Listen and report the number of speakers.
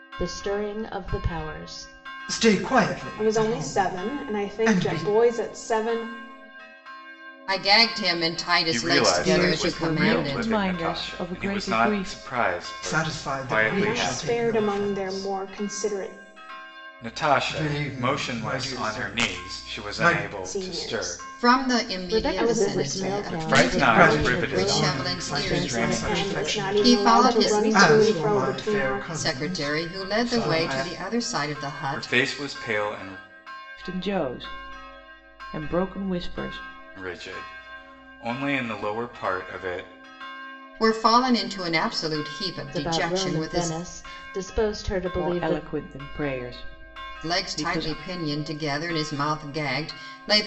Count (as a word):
six